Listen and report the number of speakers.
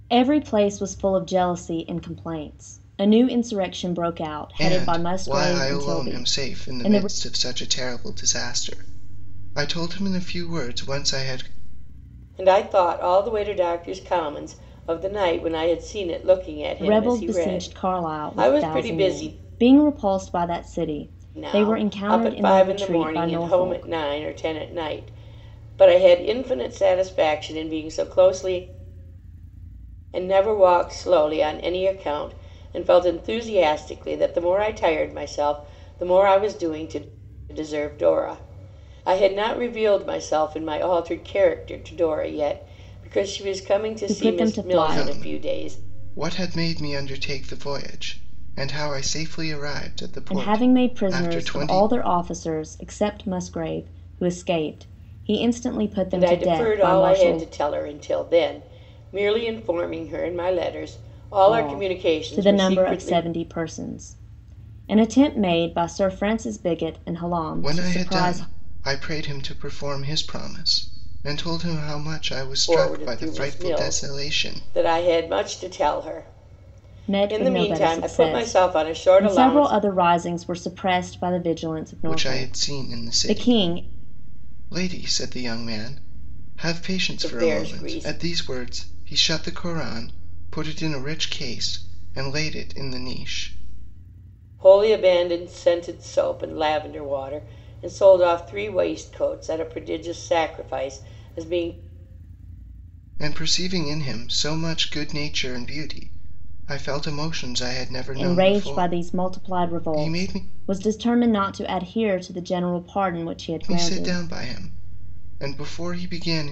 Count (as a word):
three